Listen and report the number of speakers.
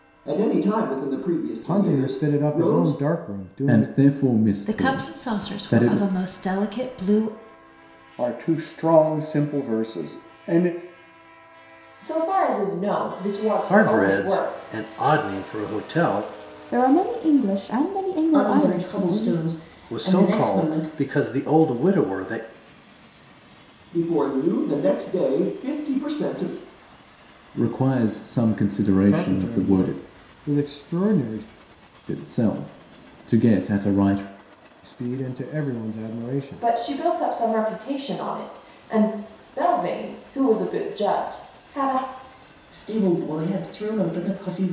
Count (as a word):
nine